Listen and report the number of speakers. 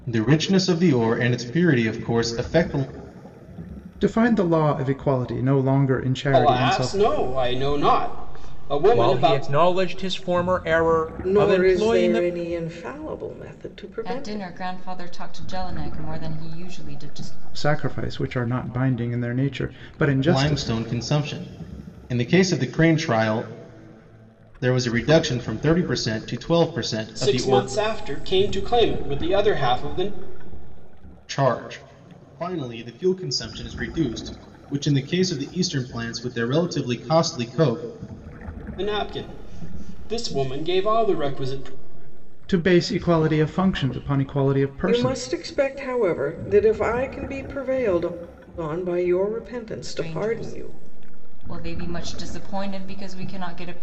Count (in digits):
6